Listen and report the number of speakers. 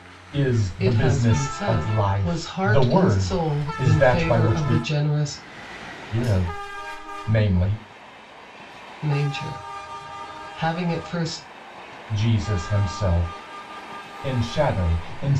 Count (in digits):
2